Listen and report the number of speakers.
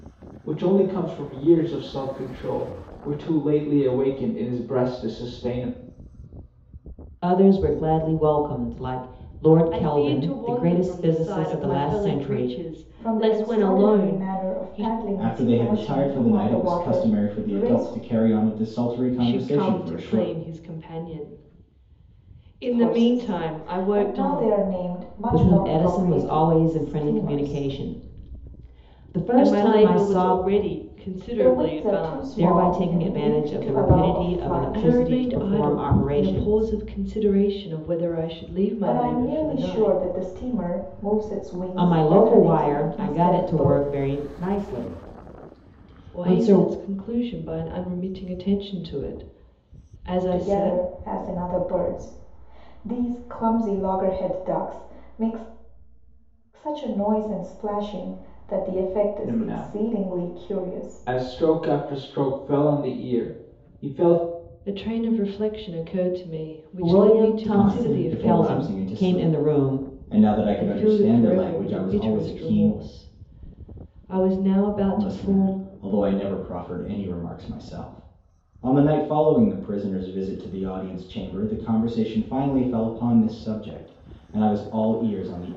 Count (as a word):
five